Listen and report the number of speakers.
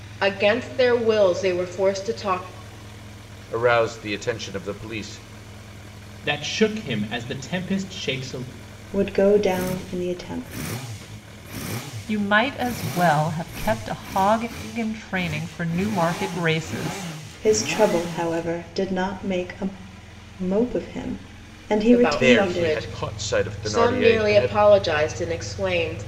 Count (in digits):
5